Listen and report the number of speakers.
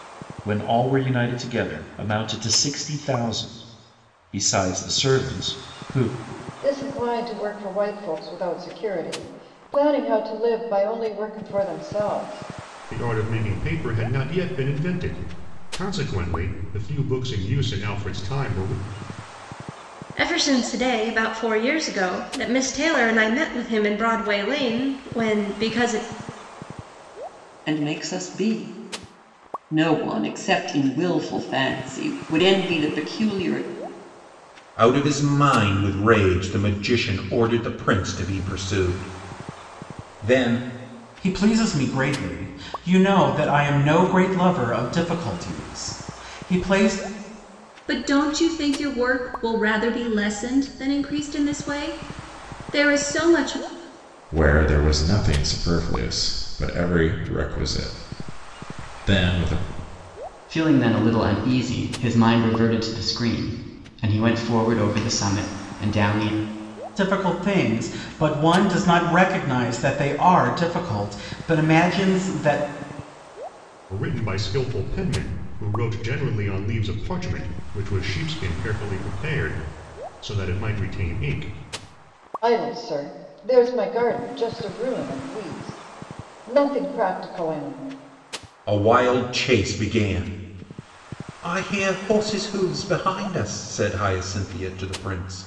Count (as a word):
ten